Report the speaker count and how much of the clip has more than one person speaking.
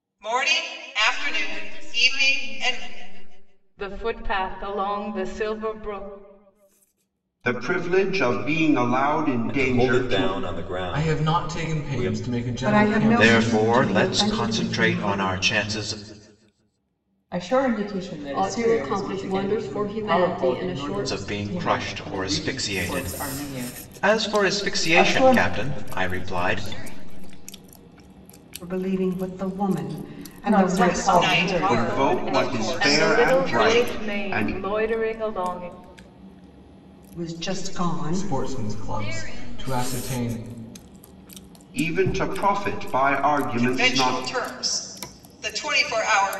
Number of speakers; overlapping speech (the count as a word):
ten, about 46%